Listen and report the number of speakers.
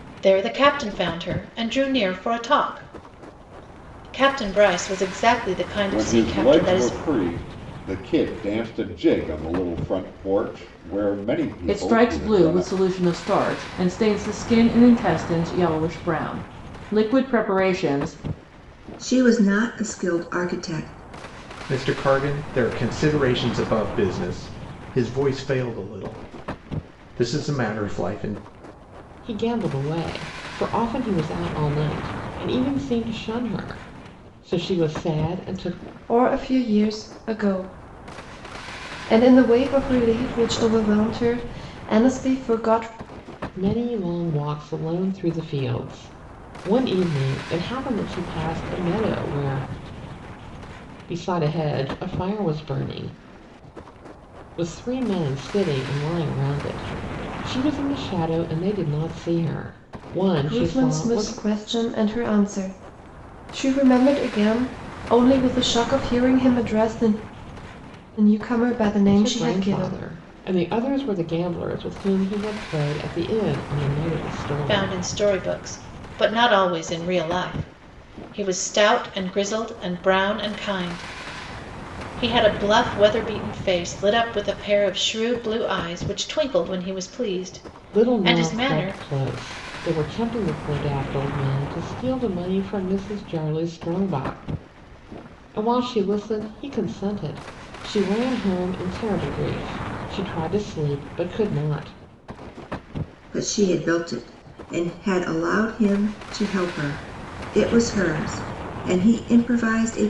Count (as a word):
seven